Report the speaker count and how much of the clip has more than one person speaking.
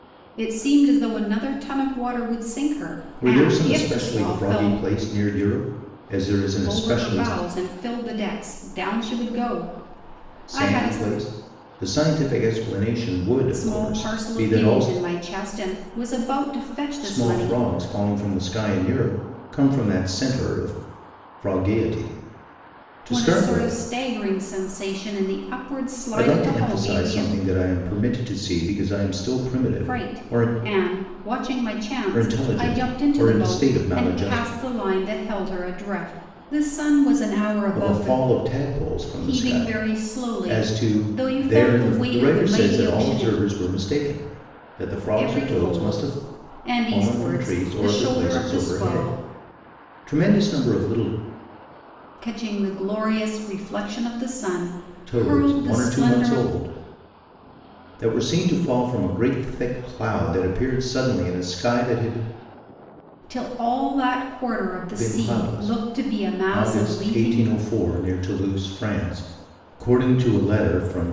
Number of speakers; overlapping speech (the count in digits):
2, about 31%